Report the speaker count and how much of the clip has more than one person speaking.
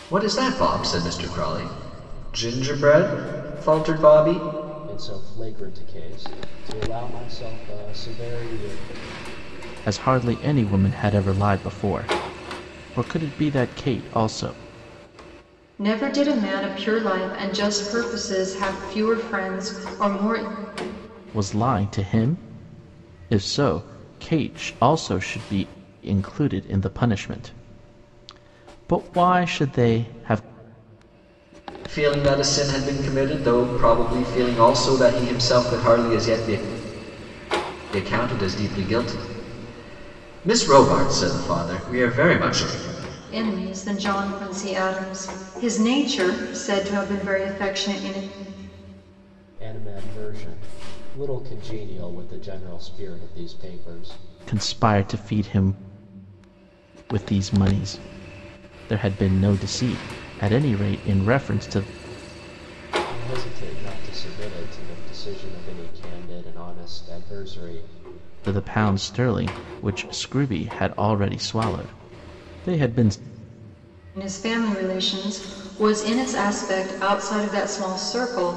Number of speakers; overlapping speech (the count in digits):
4, no overlap